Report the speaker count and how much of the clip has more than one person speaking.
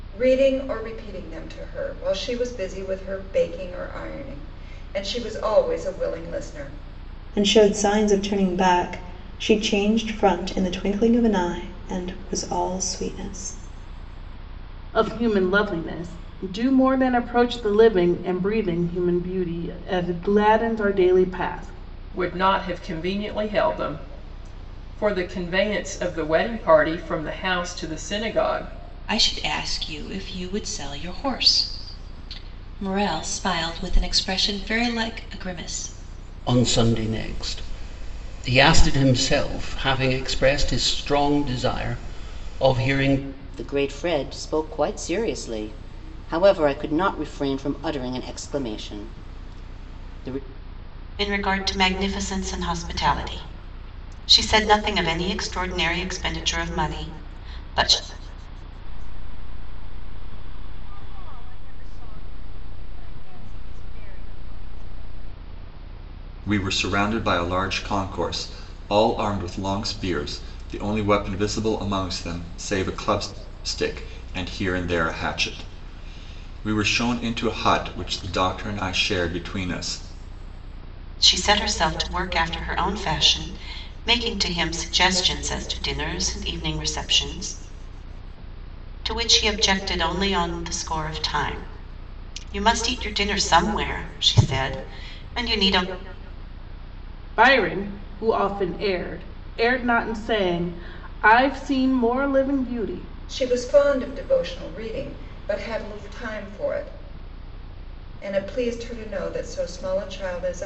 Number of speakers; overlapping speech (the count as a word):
ten, no overlap